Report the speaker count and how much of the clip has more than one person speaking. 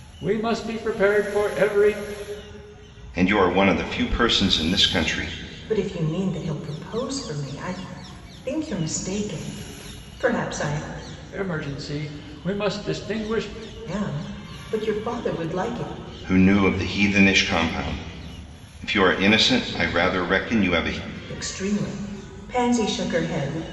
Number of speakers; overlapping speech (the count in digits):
3, no overlap